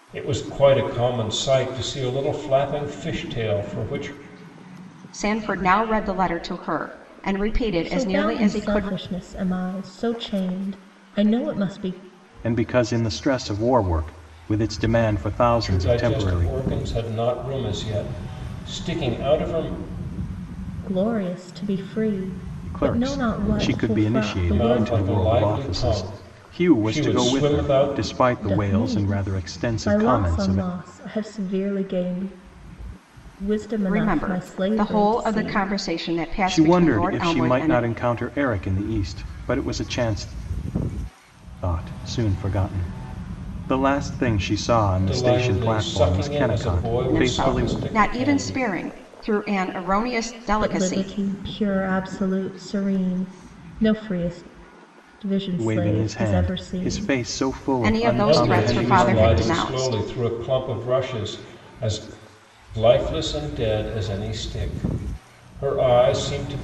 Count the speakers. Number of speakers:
4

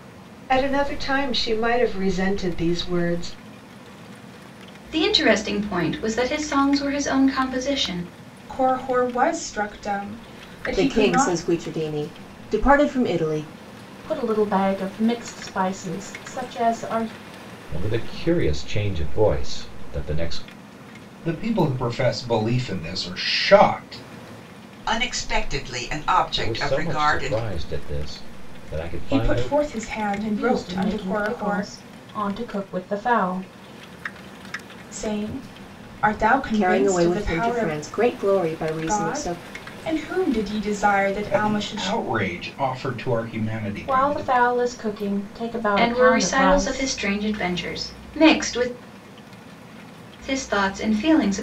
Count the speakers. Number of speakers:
8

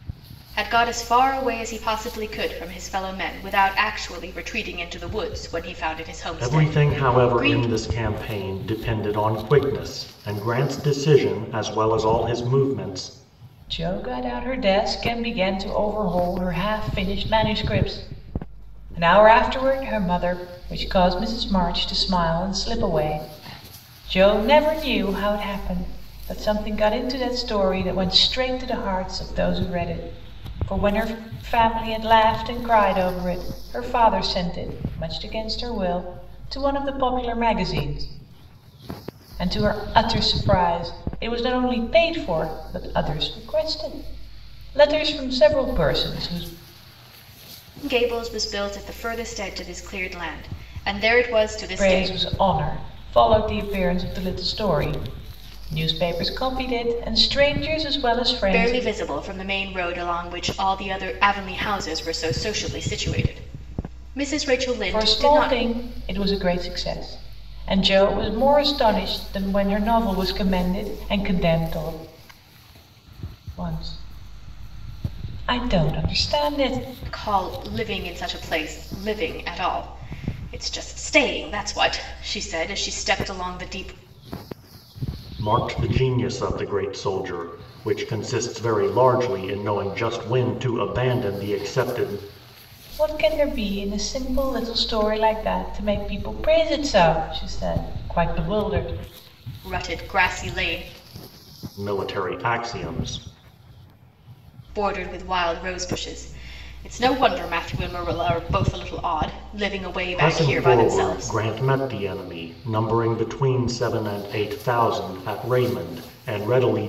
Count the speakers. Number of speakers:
3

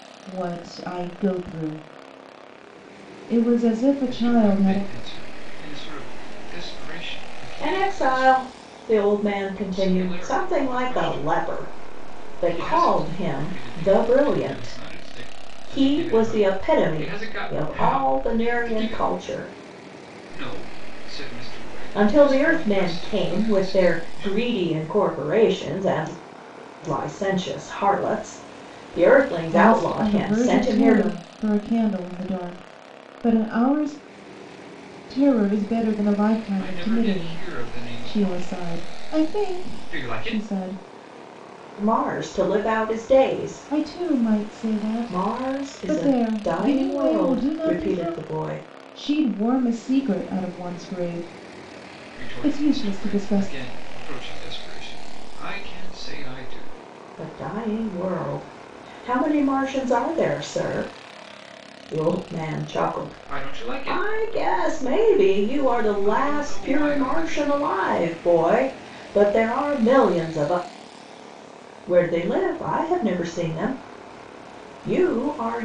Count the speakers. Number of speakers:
3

